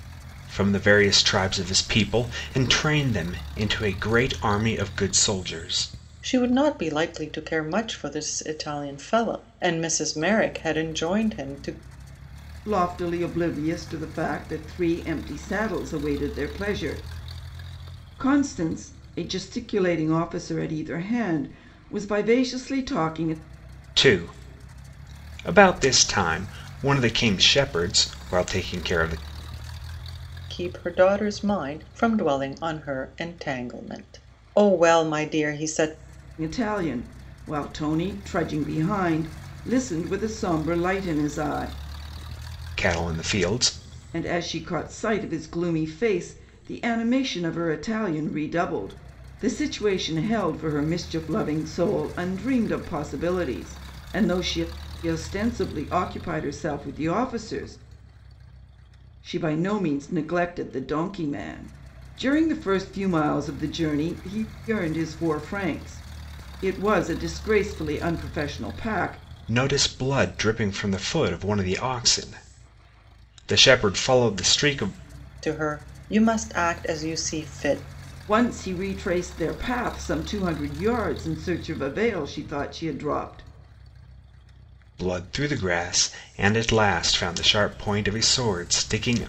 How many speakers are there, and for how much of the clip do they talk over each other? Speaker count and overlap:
three, no overlap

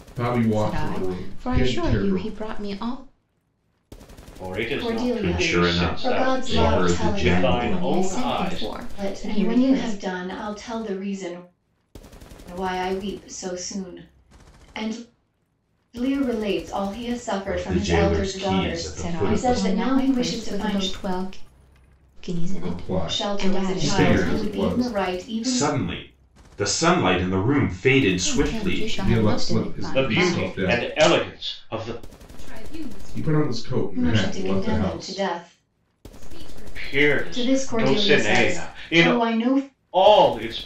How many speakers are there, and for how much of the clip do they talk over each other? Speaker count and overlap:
six, about 51%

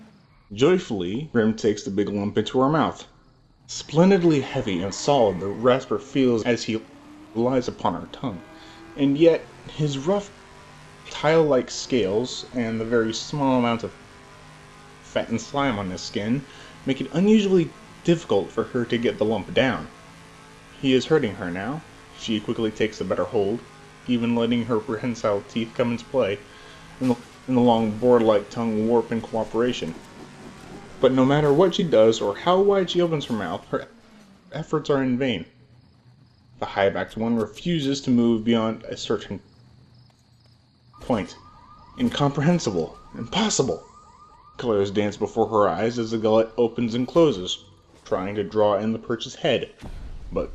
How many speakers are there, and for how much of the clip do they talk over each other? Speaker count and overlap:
one, no overlap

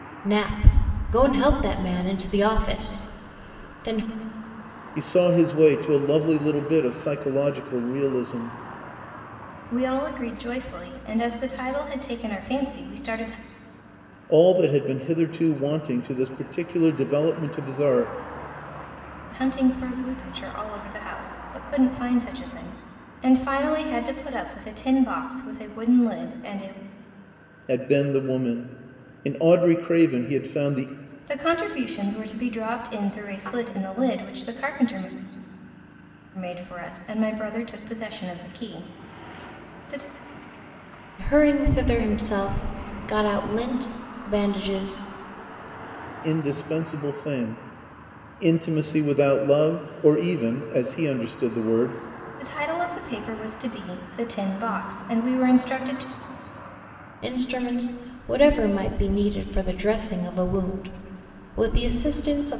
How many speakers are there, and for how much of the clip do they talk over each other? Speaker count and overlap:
three, no overlap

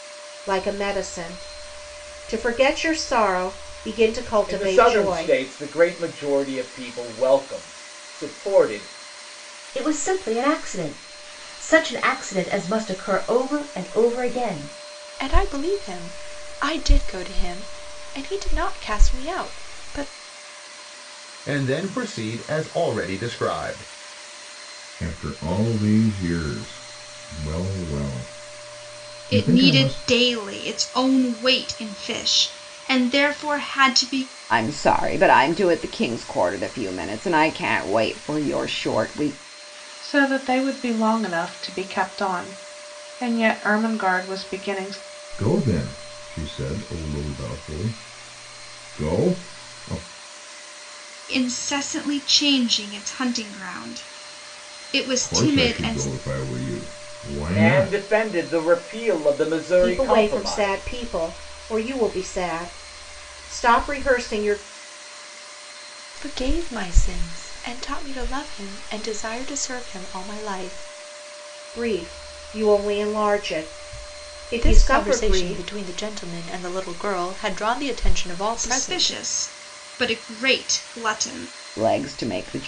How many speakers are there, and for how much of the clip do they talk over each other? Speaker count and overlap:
nine, about 7%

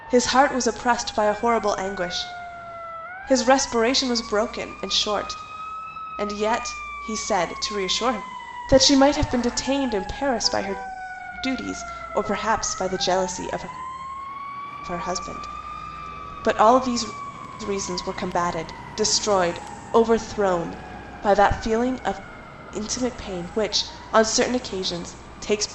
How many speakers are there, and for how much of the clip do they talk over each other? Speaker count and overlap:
one, no overlap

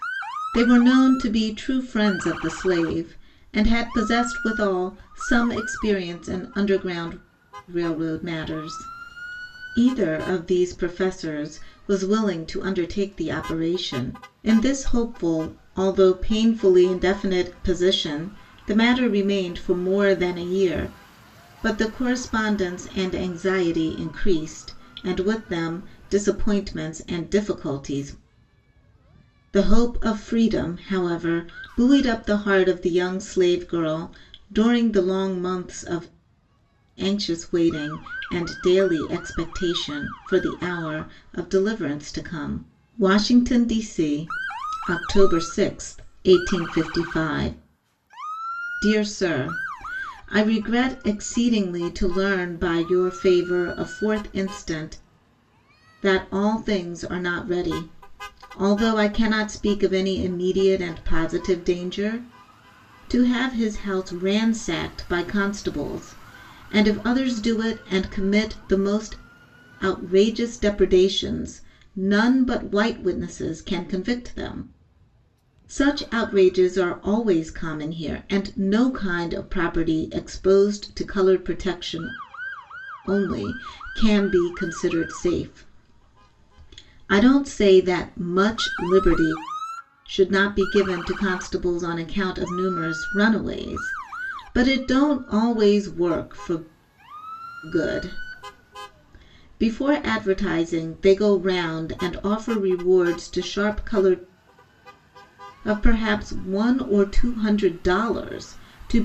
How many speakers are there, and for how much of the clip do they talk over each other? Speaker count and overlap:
one, no overlap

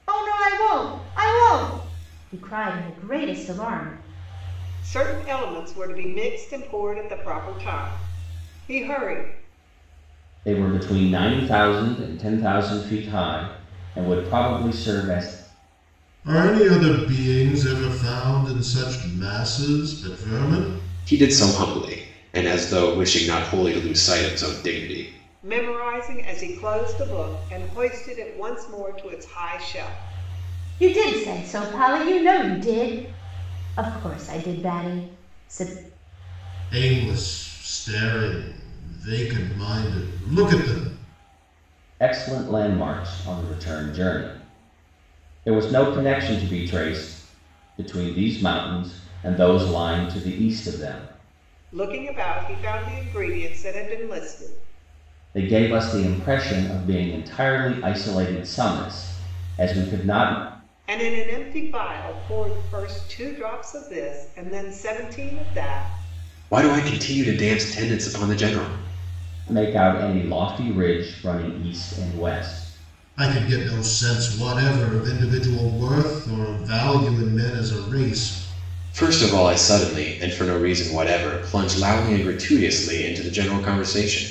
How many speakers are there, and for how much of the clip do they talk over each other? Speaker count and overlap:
five, no overlap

